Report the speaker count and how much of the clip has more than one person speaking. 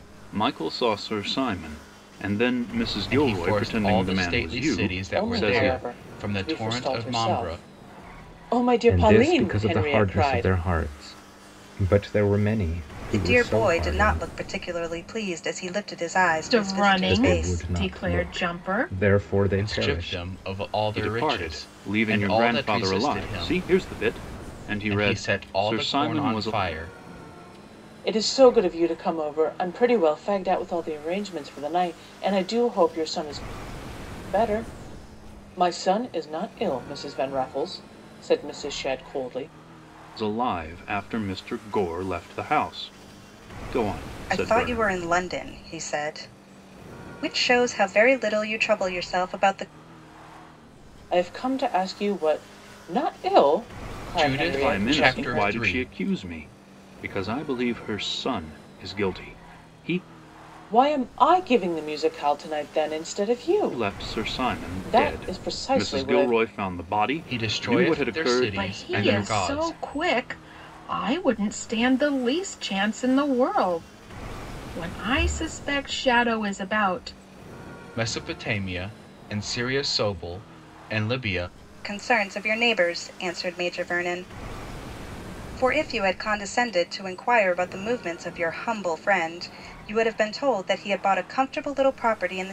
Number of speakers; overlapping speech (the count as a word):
six, about 25%